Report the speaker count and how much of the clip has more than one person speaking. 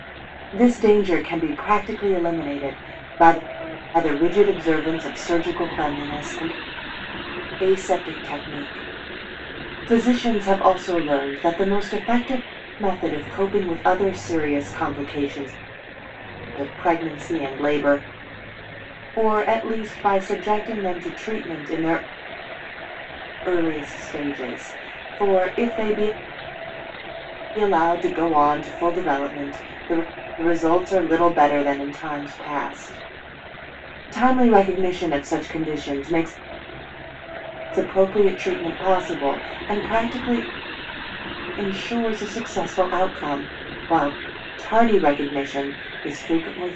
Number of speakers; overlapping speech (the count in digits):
1, no overlap